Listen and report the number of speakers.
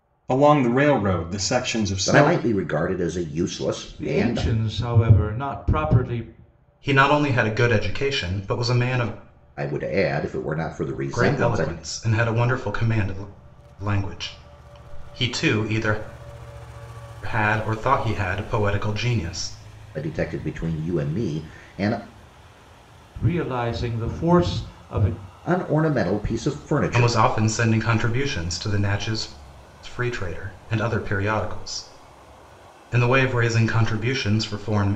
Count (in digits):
4